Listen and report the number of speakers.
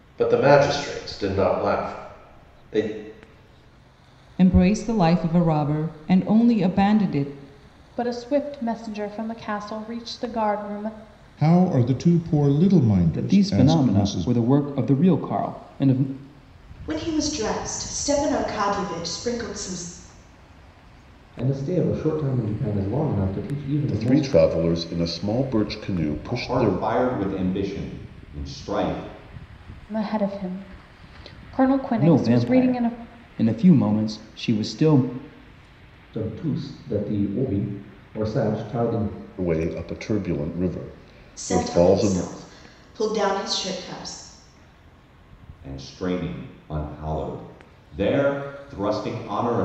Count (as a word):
nine